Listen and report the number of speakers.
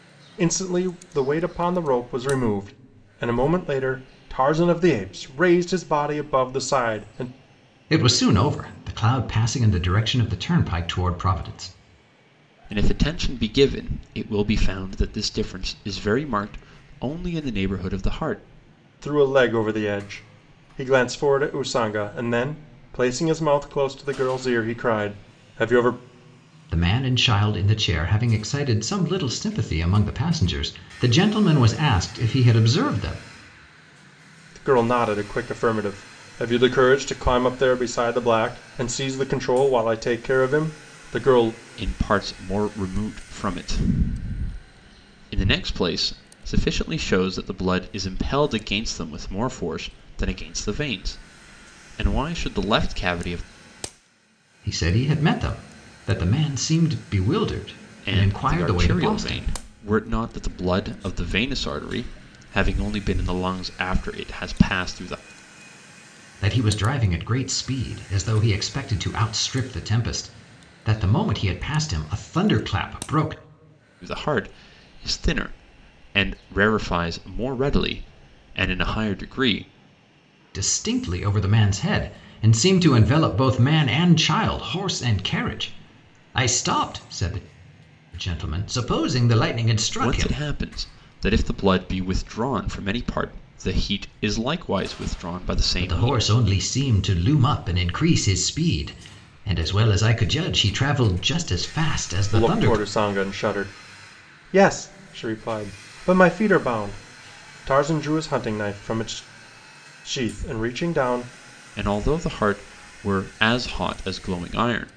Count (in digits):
3